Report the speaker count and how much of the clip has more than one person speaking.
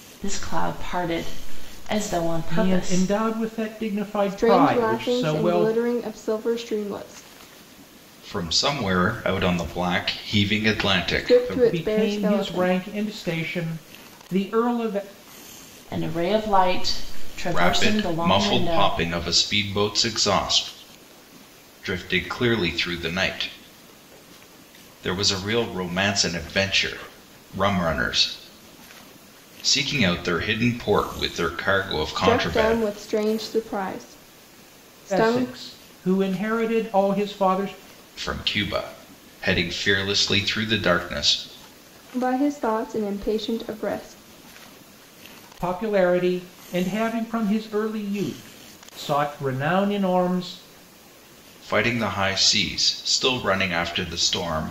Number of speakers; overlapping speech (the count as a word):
four, about 11%